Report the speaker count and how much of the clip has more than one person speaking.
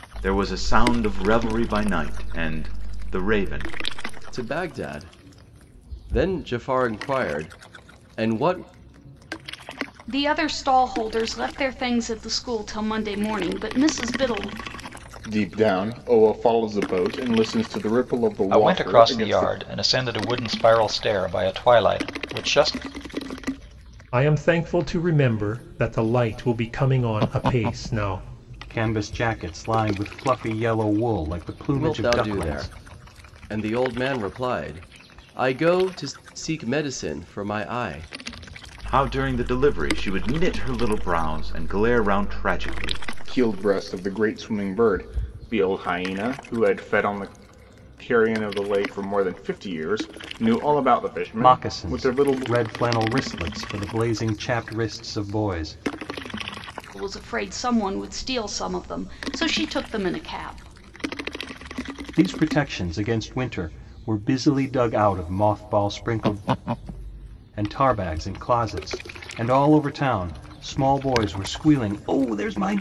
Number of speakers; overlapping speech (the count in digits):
7, about 4%